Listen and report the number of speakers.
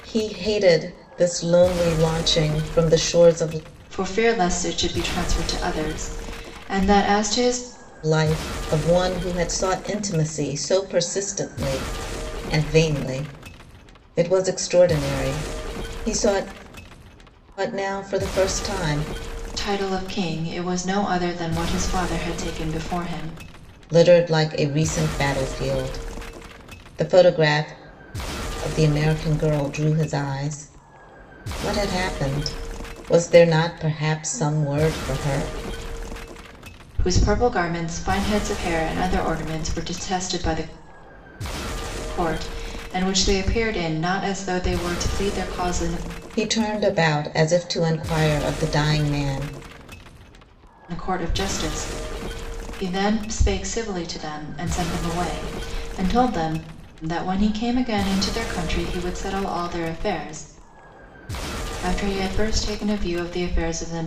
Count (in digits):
2